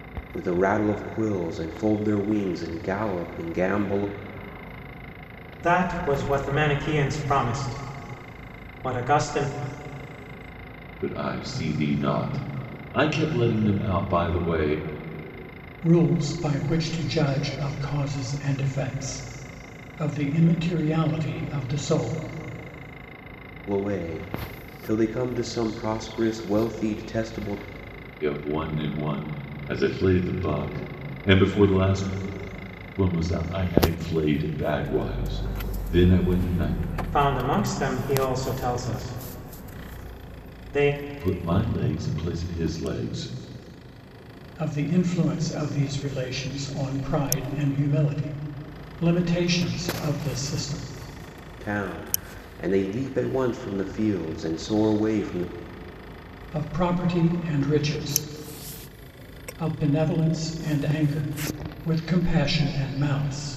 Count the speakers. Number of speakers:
four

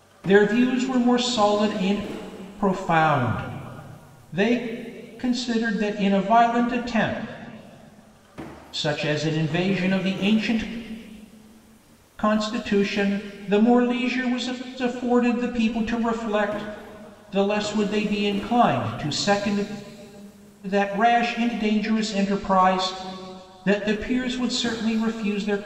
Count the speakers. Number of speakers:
one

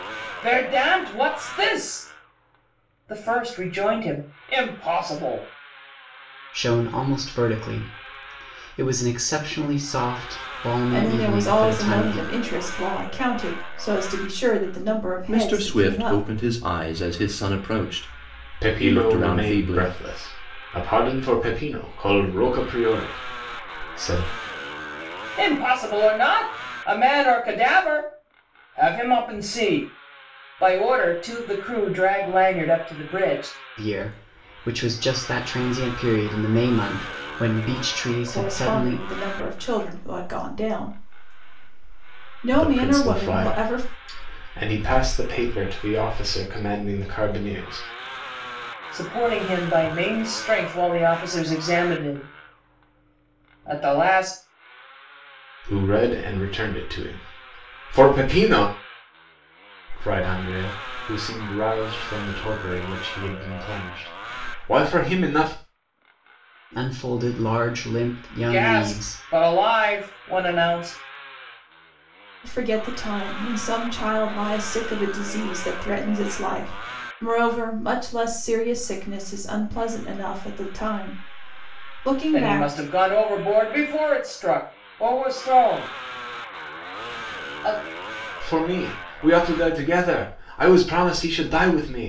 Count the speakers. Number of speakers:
five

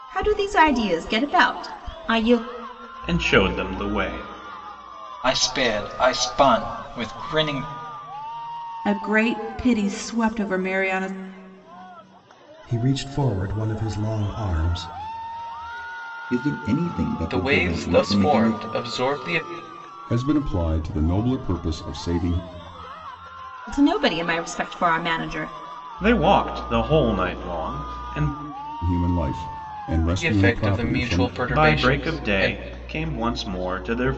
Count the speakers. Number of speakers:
eight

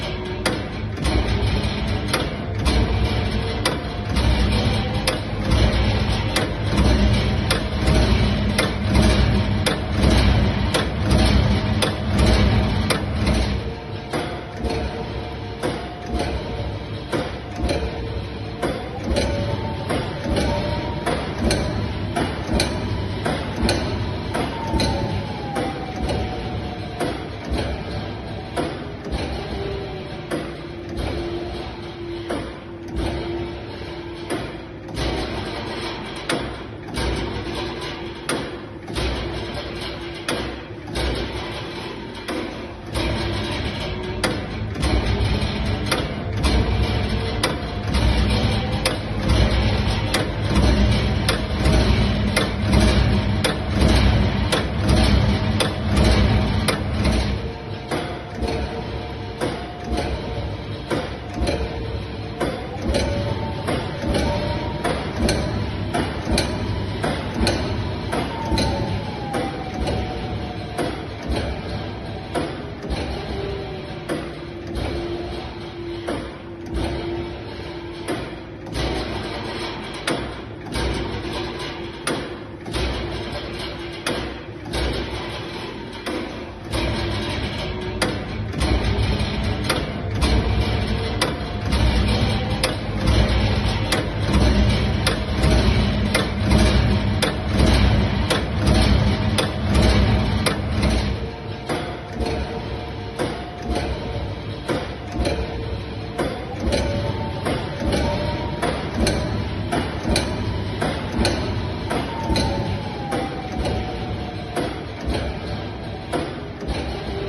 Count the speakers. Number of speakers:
zero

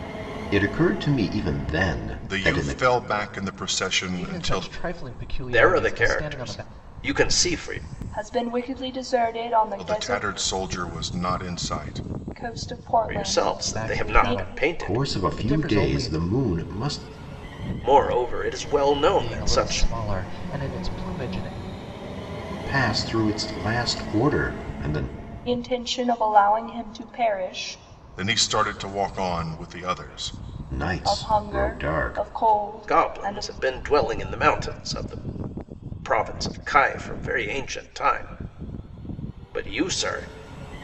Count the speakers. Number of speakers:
five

